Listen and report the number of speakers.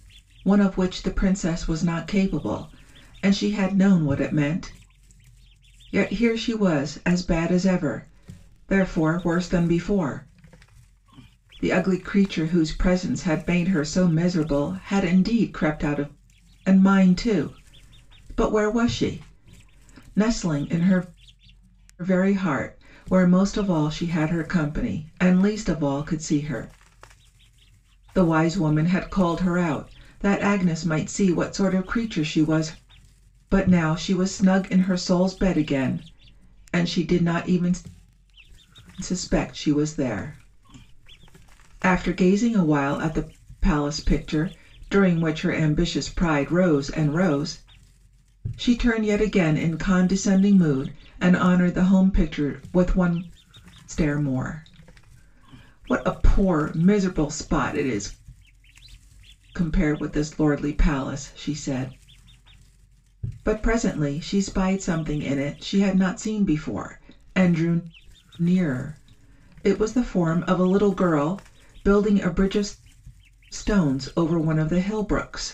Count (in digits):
1